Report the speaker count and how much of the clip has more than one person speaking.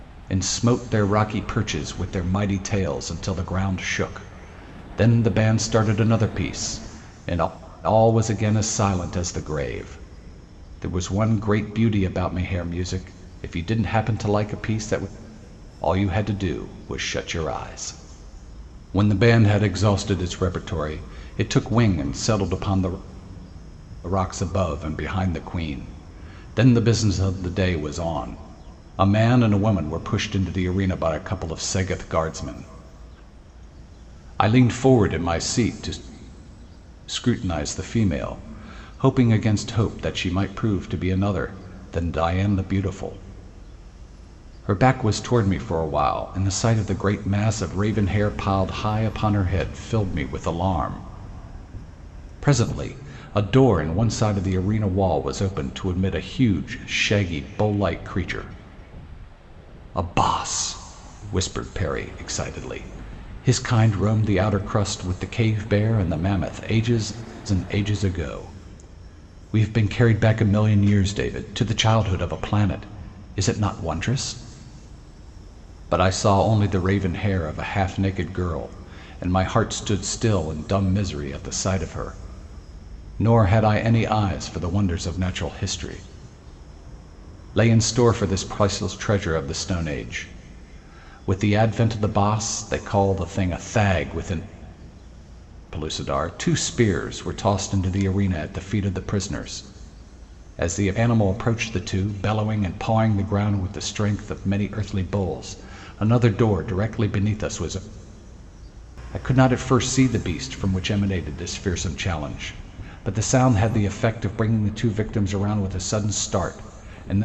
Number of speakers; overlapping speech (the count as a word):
one, no overlap